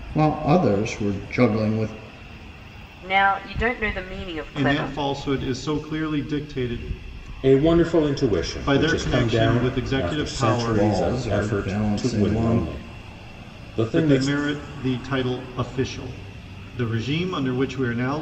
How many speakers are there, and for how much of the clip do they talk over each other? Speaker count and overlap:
4, about 26%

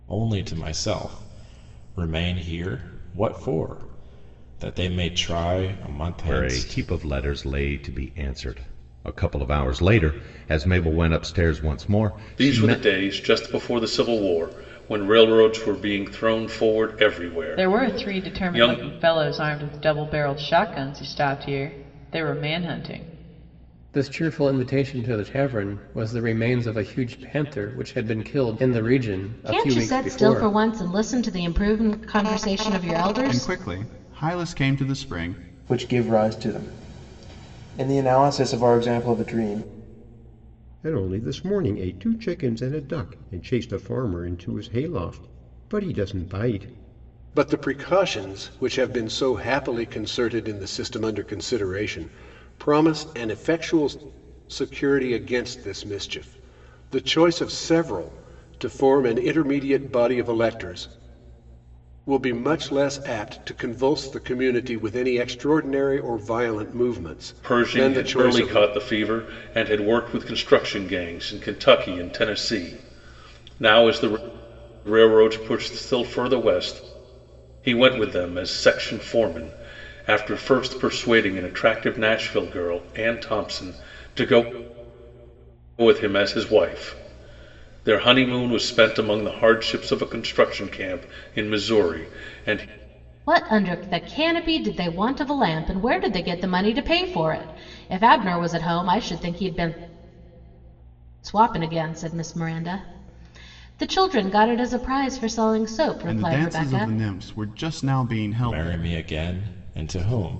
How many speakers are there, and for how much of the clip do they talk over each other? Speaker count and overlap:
10, about 6%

